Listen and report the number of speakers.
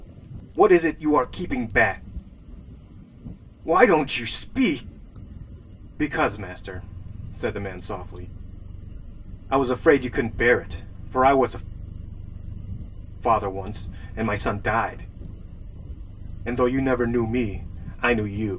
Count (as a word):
one